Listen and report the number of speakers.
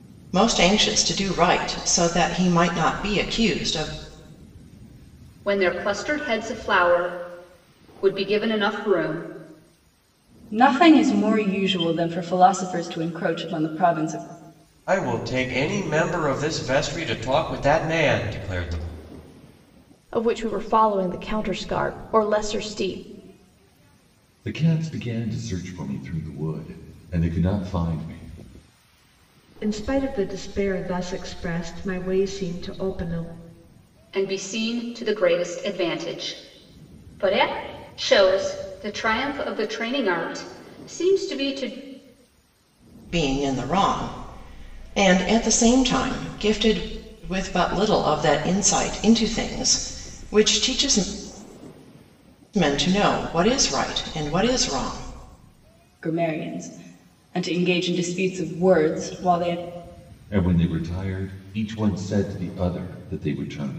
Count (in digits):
7